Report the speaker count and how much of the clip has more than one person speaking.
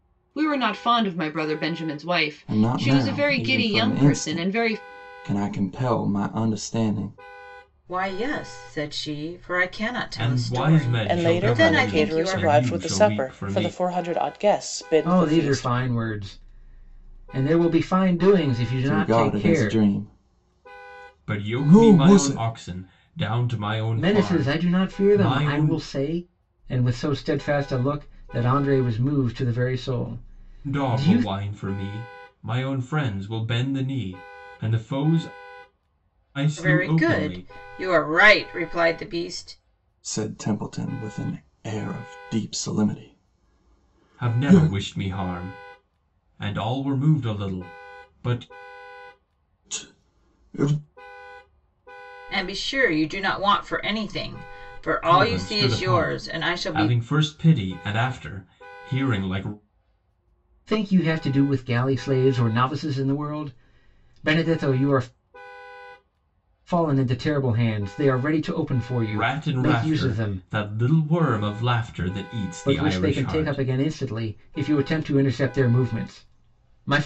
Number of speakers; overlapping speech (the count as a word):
six, about 23%